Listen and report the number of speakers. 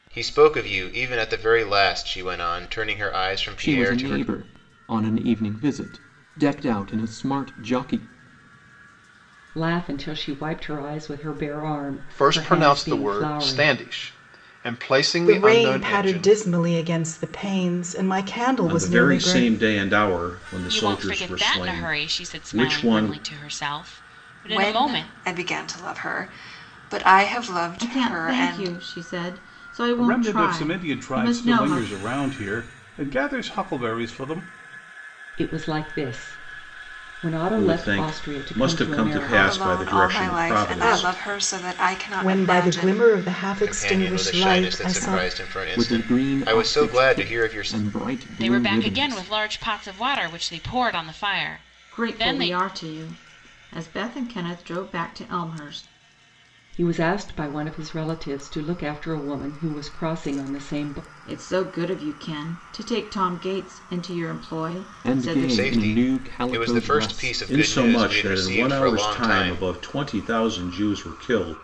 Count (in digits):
10